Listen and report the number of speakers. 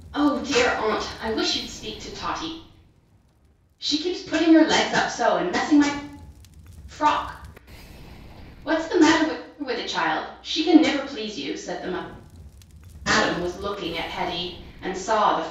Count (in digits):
1